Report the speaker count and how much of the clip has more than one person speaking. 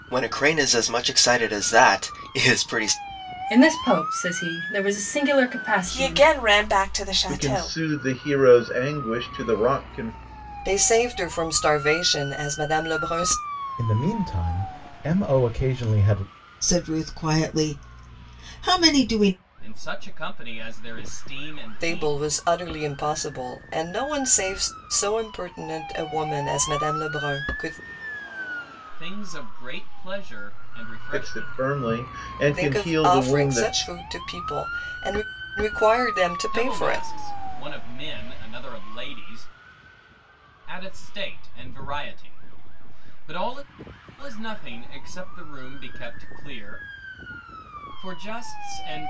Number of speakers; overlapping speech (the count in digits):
8, about 8%